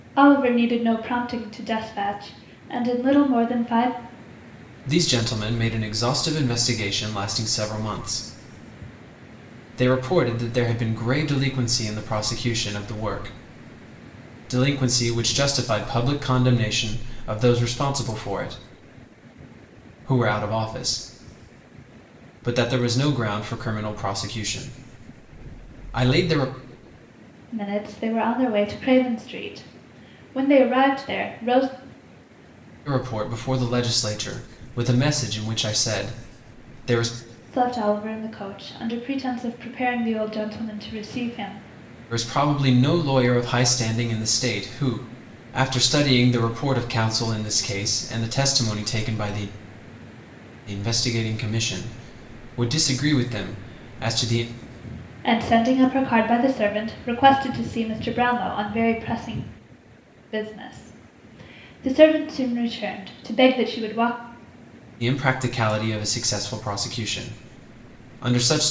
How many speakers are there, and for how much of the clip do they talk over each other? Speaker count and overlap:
2, no overlap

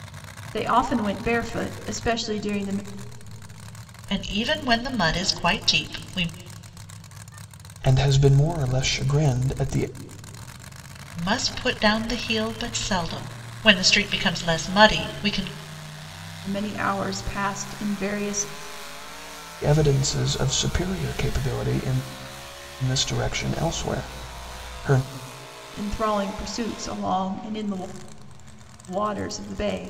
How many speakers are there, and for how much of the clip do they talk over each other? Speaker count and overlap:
3, no overlap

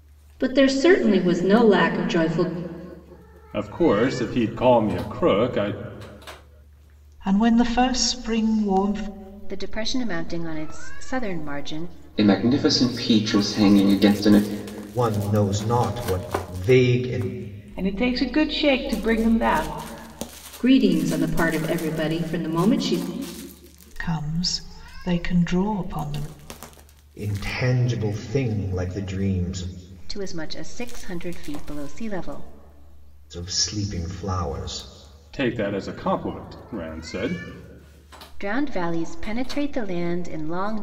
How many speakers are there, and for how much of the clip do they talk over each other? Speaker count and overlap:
7, no overlap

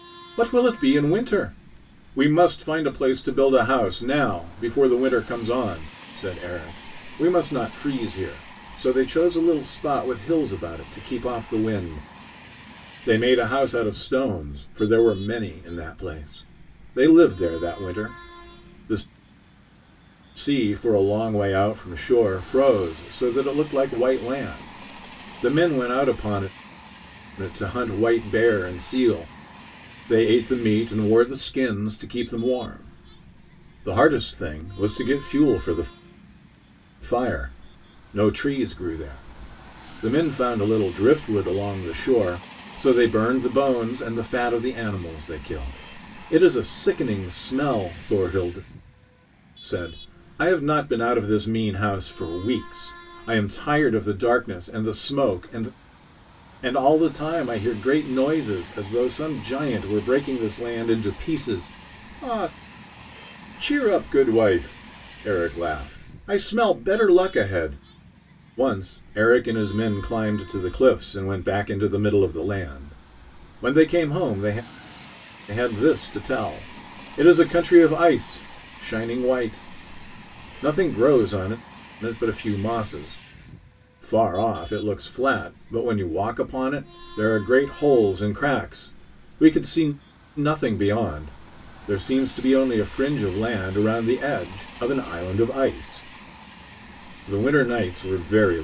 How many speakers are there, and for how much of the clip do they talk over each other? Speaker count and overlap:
1, no overlap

